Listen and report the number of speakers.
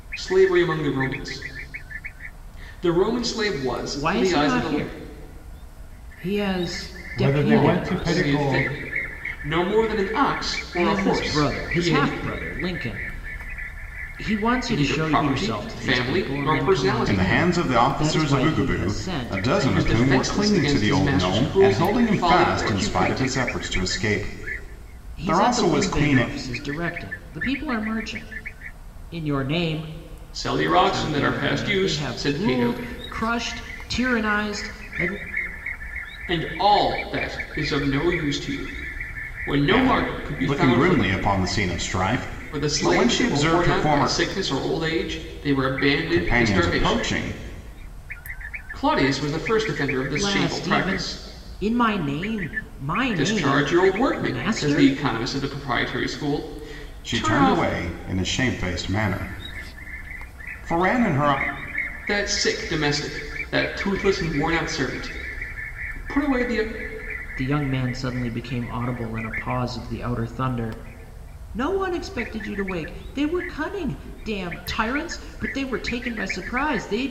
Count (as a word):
three